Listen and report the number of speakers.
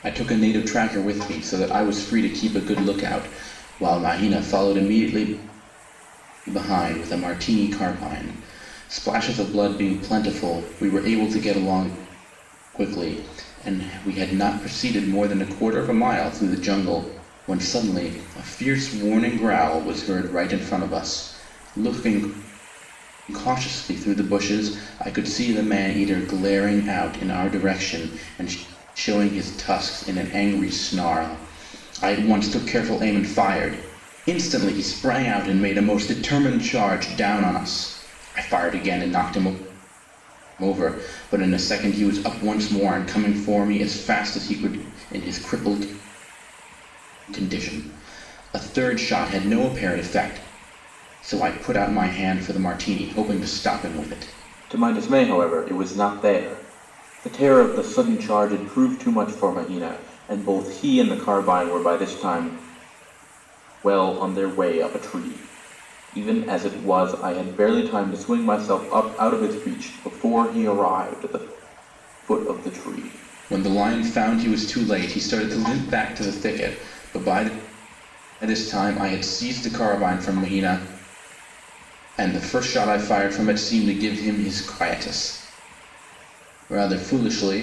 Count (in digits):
1